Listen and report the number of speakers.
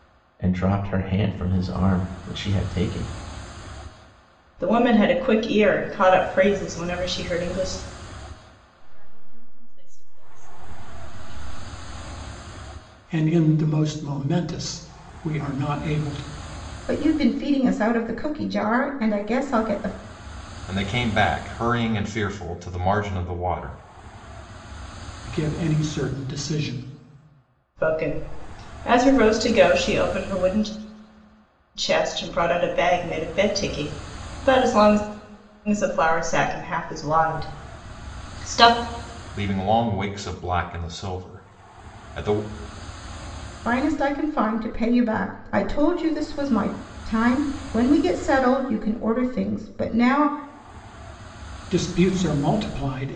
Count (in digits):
6